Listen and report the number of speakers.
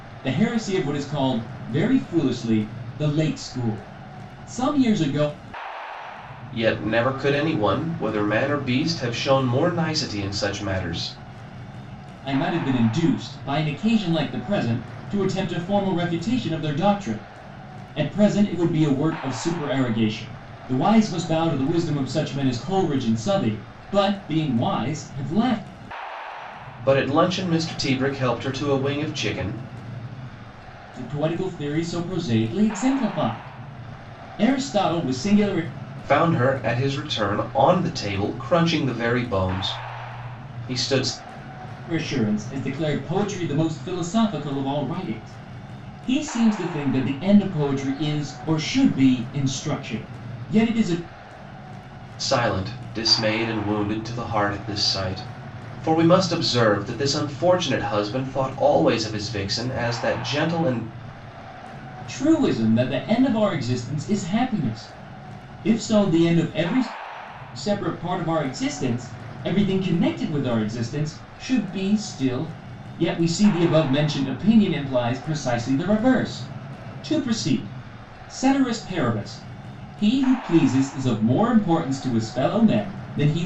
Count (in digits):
2